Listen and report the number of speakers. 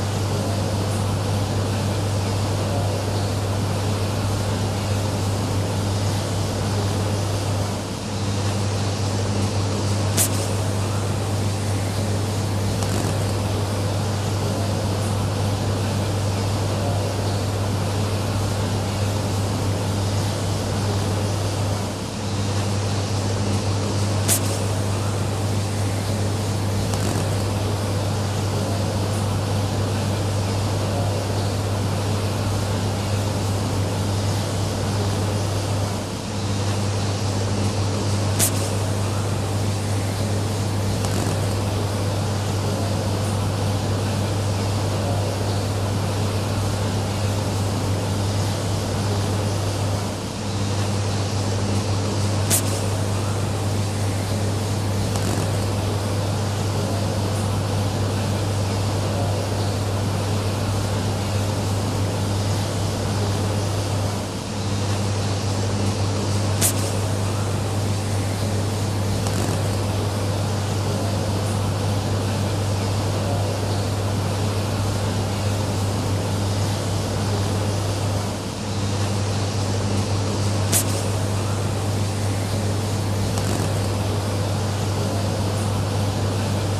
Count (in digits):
0